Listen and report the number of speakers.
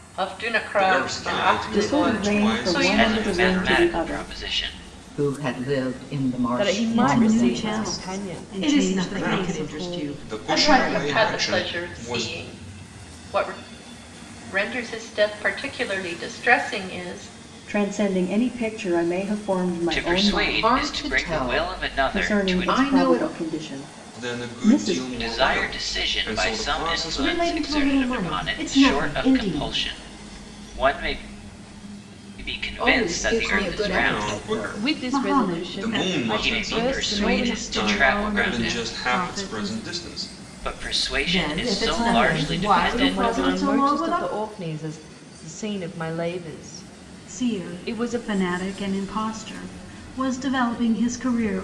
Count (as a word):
eight